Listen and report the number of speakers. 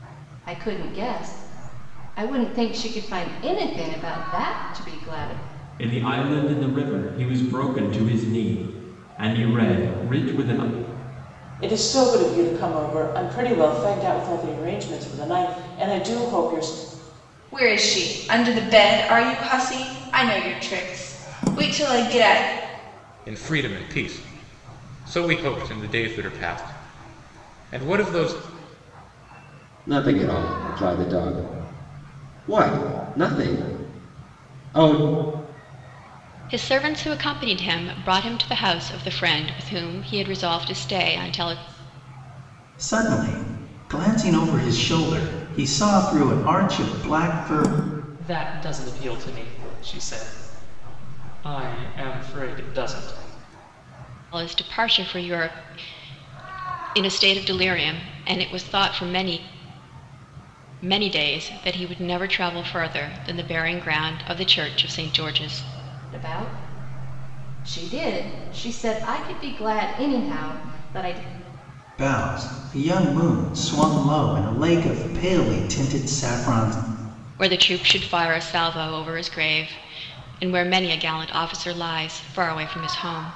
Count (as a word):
nine